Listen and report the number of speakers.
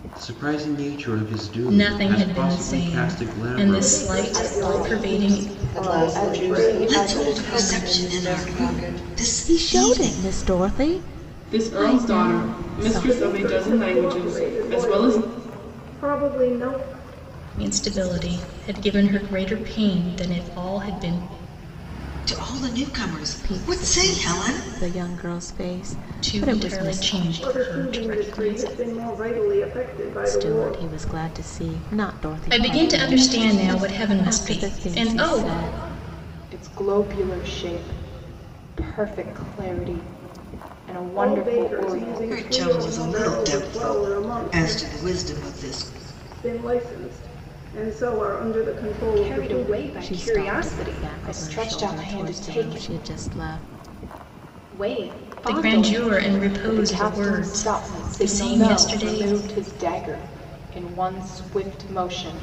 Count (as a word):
eight